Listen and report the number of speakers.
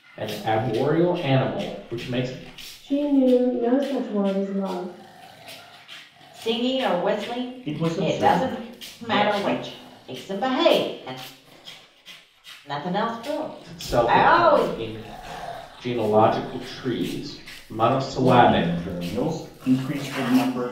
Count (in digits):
4